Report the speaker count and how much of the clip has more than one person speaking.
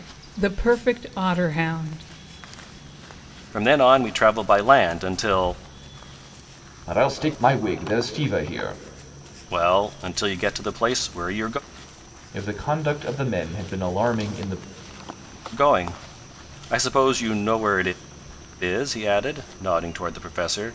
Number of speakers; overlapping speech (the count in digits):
3, no overlap